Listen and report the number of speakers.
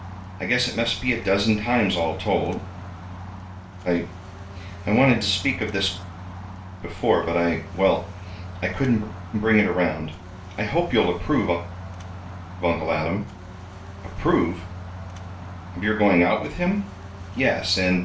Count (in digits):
1